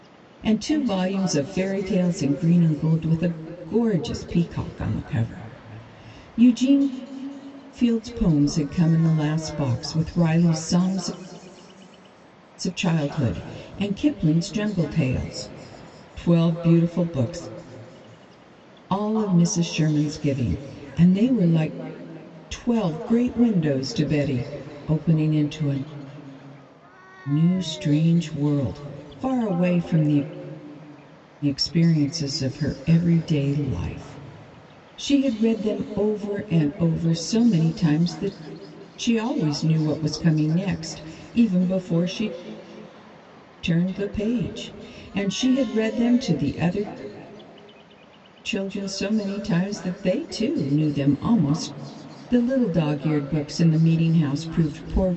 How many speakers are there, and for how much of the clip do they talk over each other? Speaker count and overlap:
1, no overlap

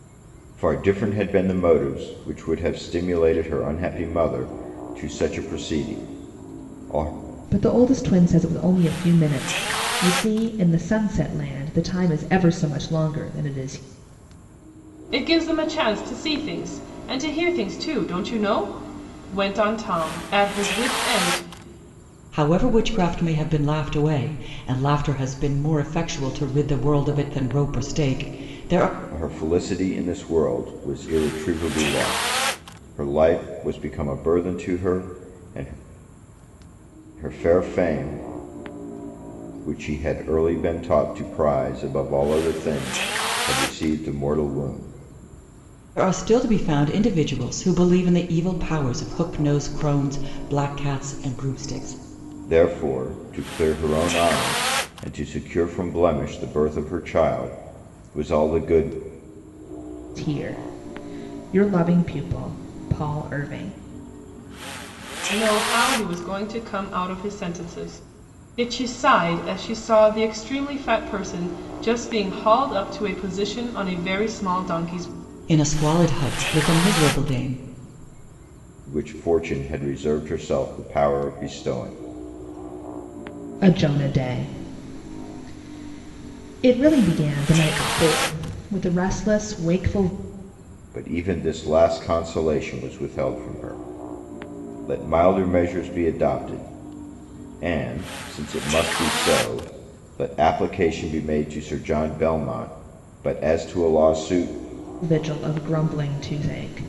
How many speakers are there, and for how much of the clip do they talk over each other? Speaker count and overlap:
4, no overlap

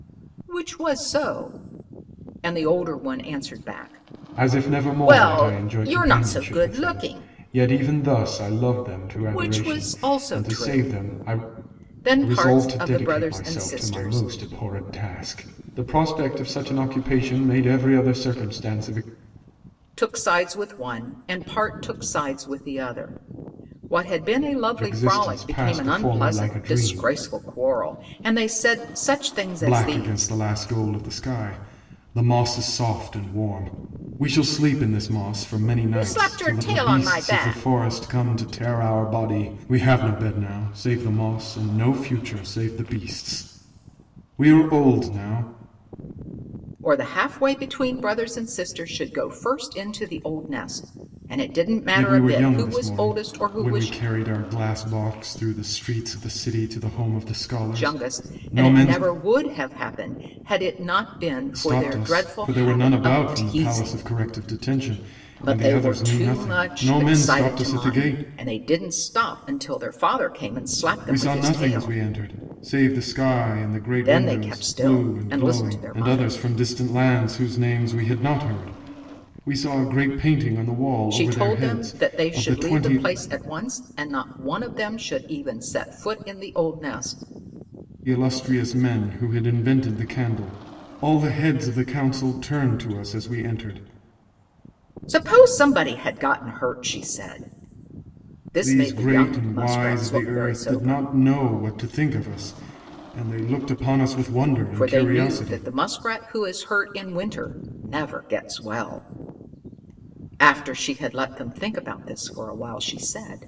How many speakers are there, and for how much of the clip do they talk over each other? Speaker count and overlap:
2, about 26%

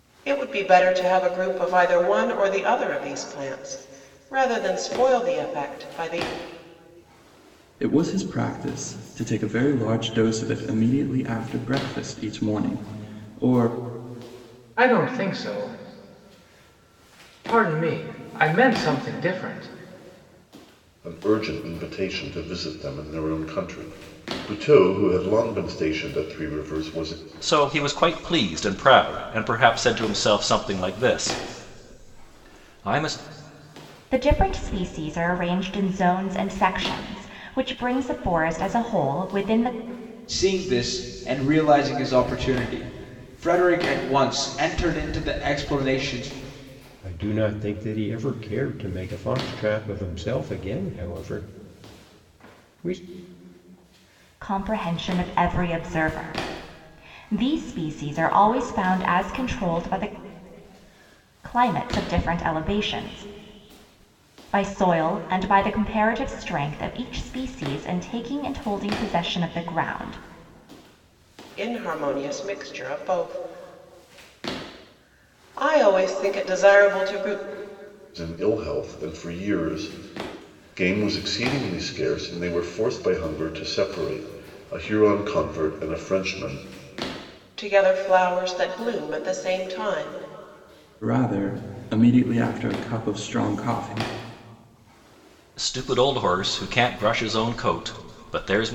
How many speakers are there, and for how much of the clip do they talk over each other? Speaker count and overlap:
8, no overlap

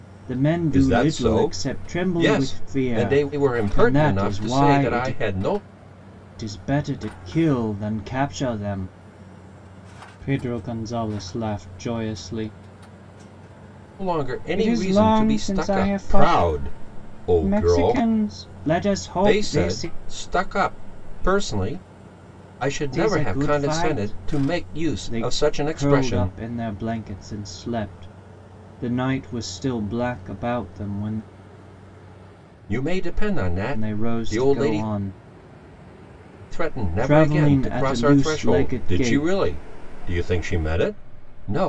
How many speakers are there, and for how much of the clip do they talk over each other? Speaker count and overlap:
2, about 34%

